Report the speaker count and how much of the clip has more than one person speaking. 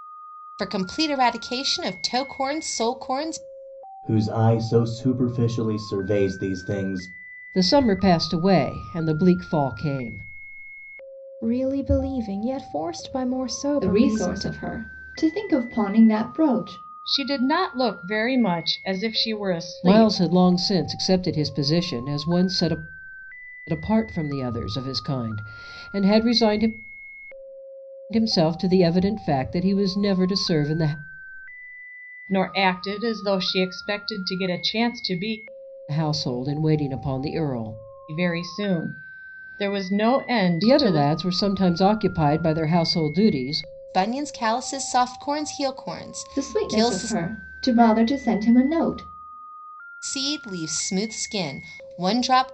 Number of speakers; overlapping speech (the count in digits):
6, about 5%